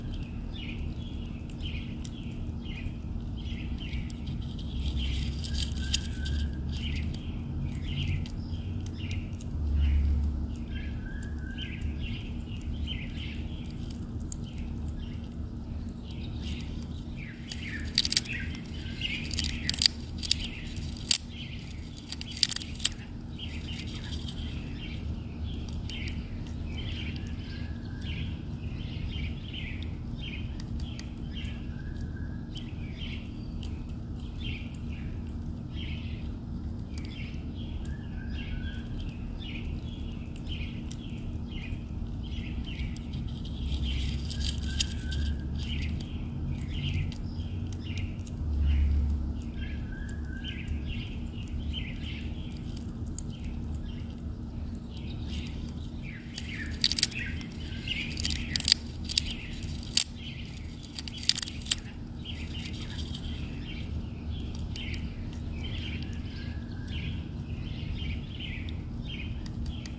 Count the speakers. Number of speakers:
zero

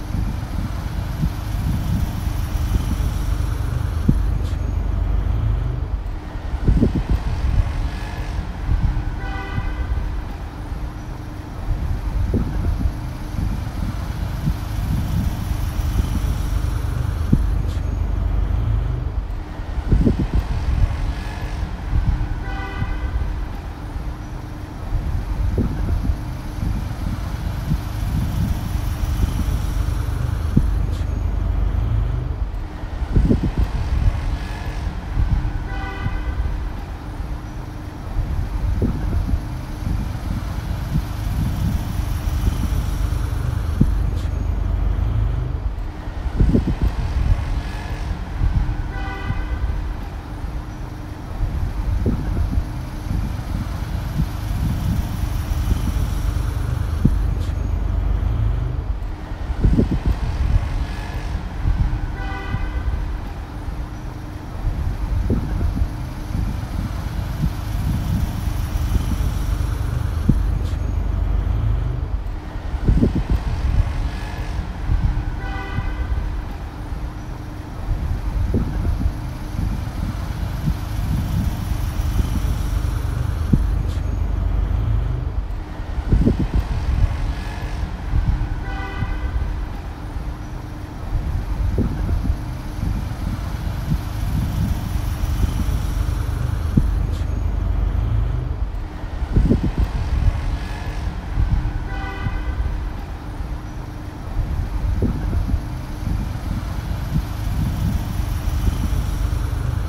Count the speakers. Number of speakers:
zero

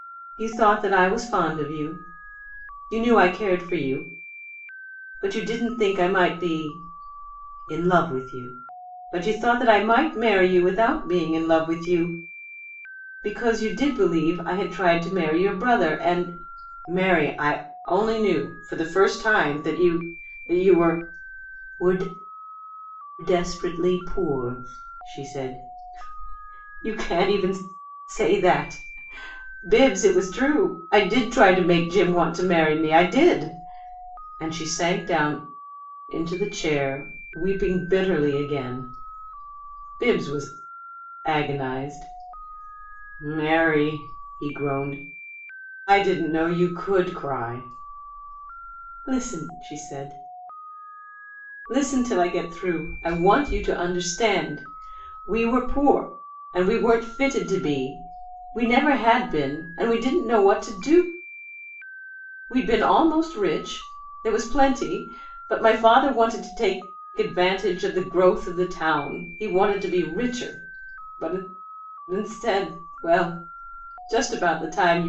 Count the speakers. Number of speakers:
one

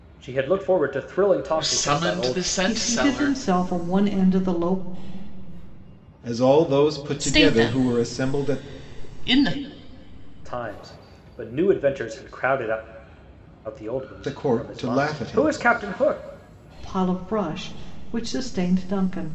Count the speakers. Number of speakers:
five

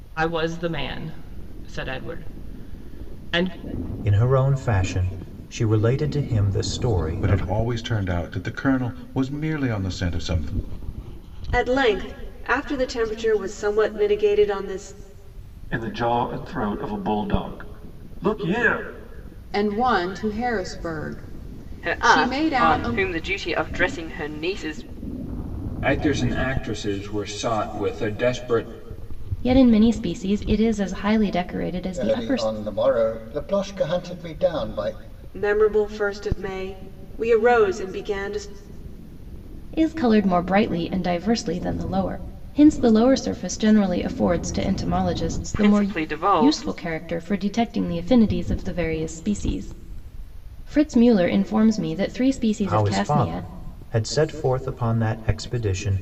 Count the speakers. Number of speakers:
ten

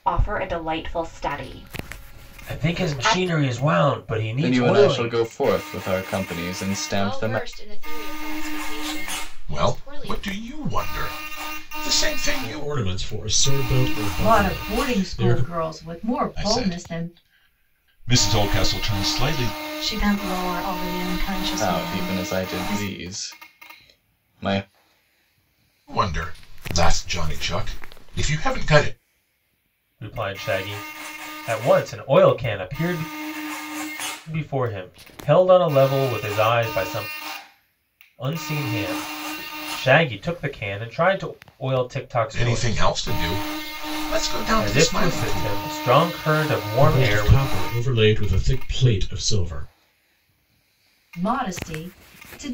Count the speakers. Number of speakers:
nine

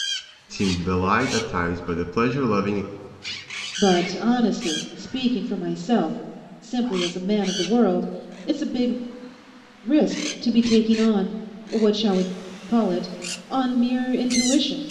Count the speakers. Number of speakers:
two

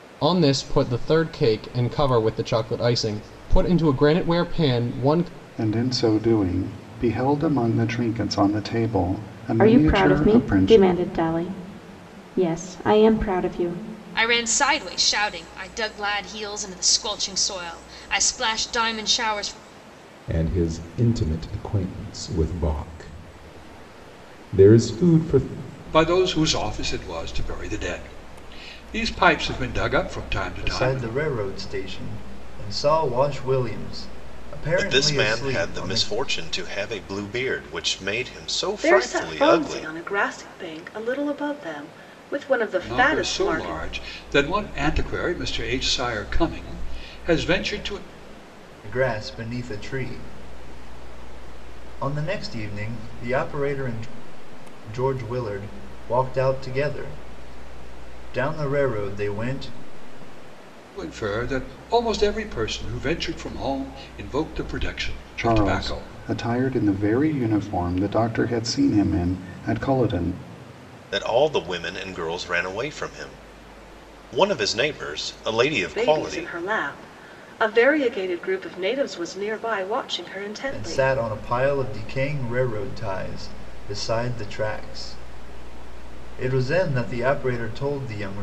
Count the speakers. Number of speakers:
nine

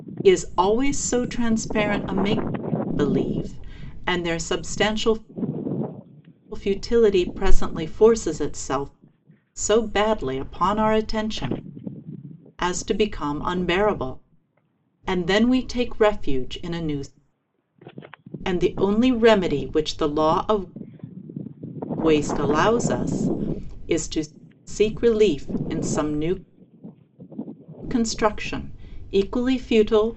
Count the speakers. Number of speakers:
one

